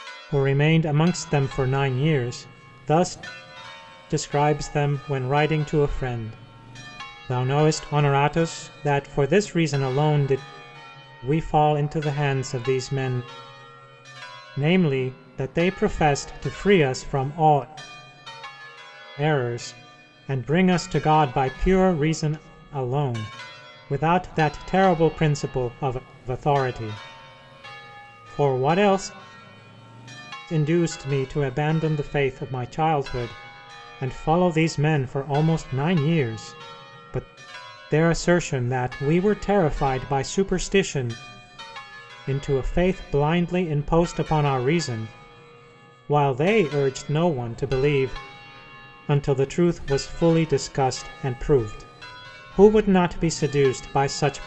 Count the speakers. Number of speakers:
1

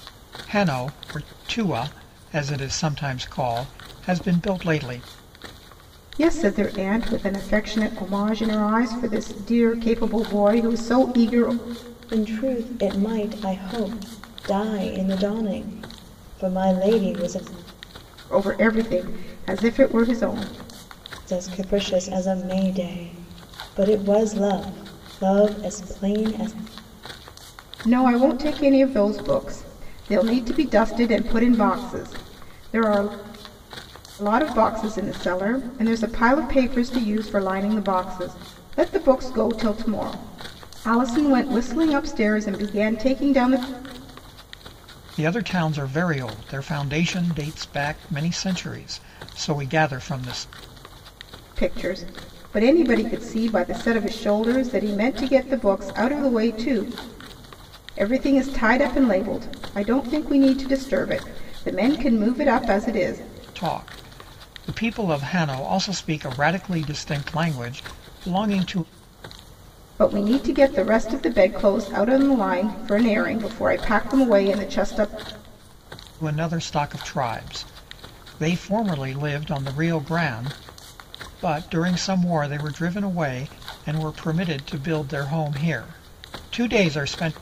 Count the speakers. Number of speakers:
3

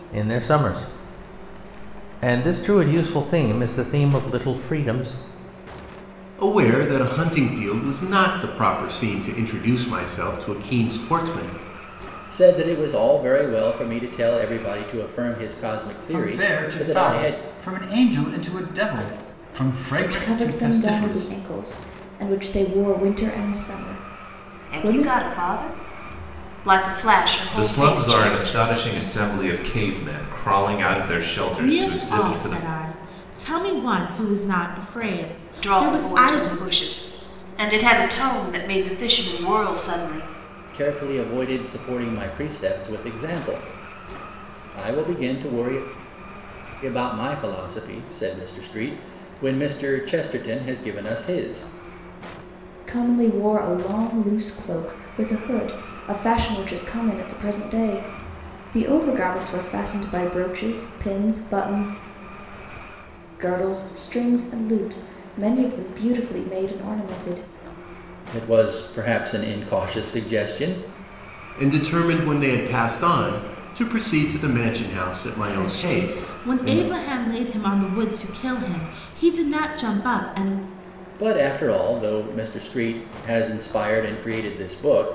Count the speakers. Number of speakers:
8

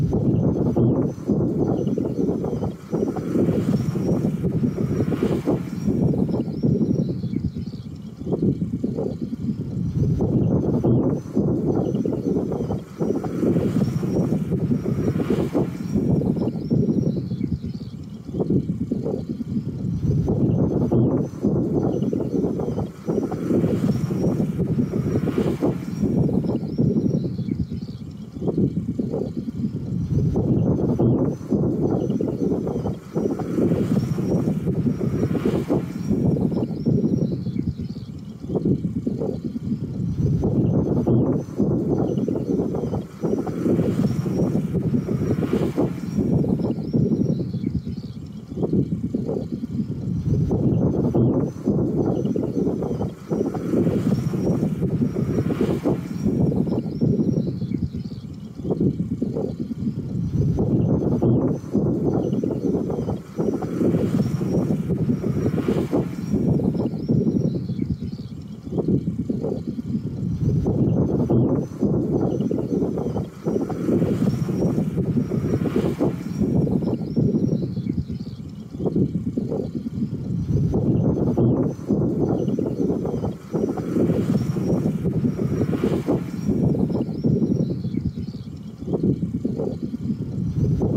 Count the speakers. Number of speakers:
0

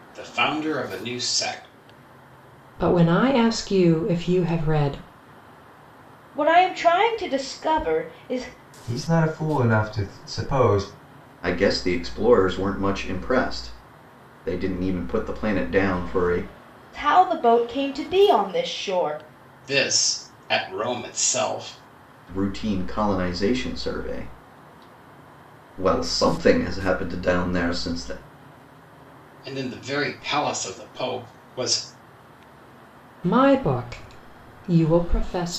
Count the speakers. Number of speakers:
5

